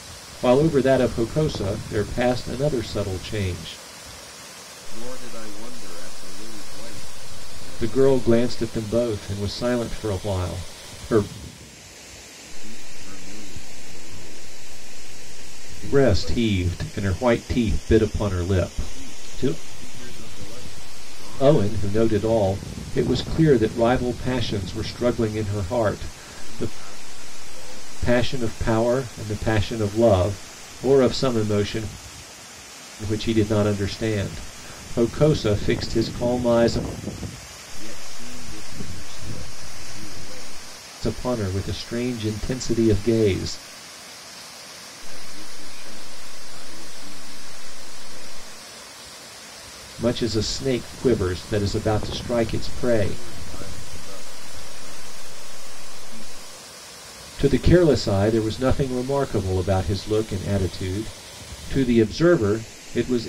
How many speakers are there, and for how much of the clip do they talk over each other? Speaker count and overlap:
2, about 7%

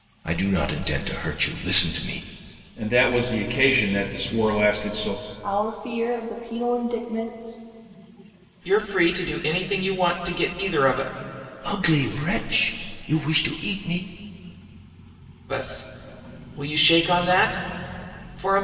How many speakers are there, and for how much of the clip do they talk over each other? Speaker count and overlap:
4, no overlap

